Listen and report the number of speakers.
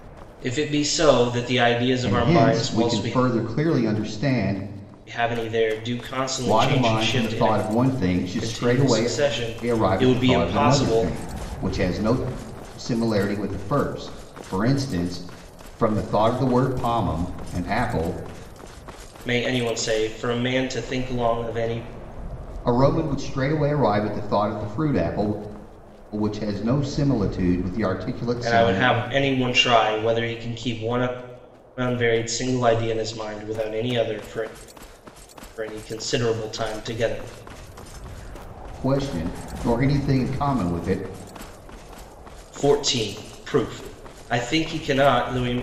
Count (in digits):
2